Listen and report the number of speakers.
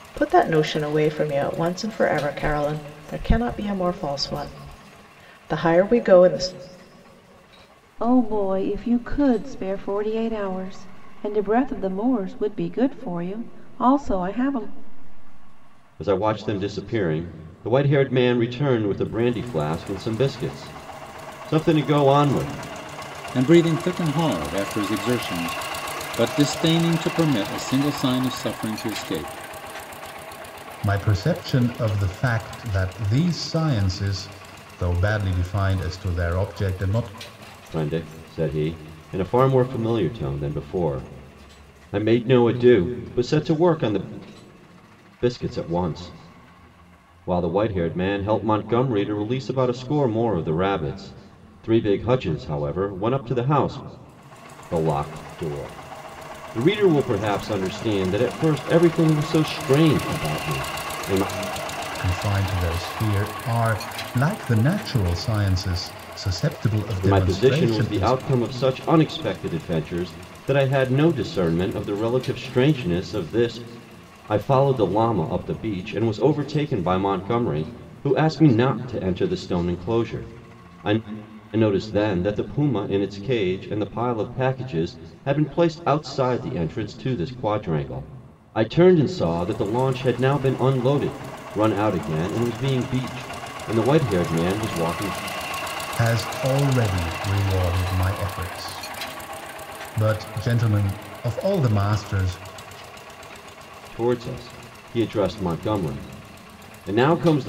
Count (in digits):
5